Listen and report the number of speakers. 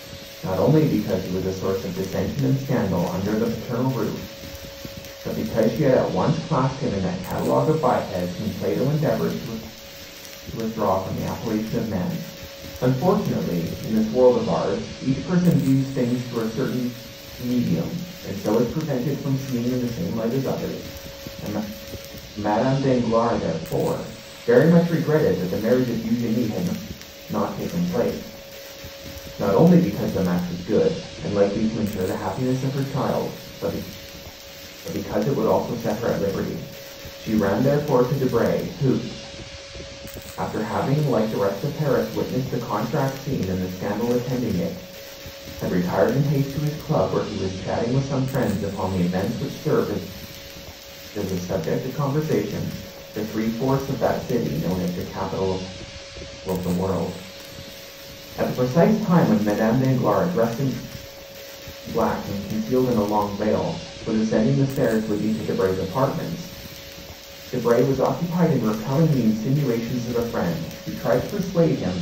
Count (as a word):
one